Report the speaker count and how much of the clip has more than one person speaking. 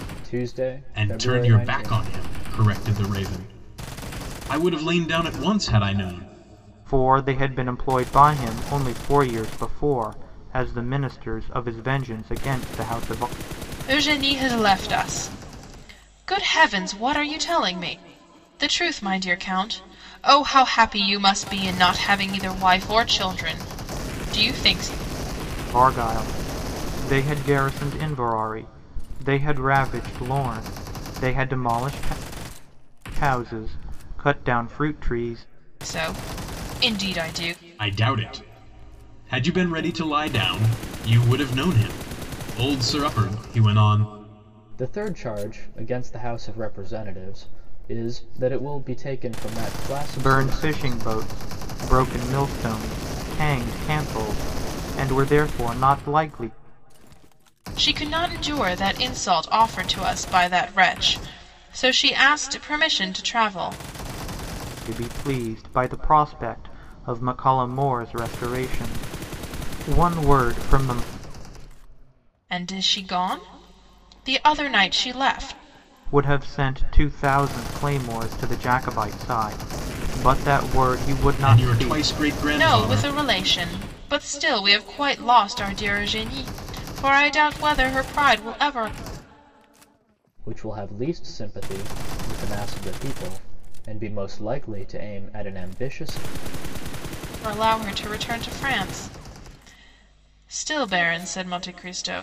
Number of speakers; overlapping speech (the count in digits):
4, about 3%